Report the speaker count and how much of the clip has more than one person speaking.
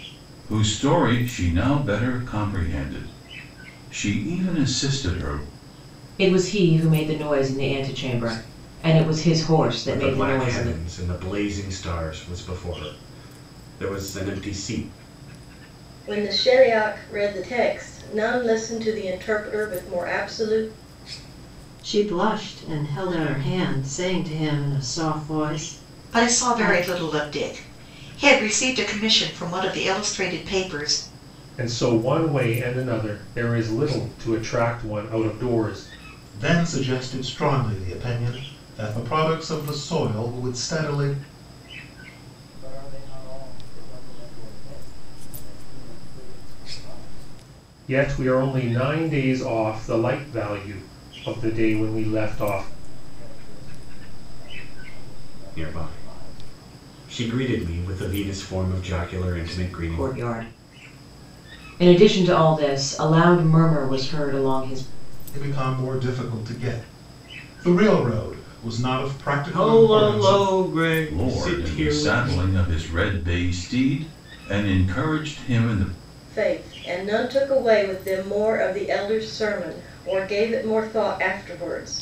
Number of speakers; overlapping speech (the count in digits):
9, about 10%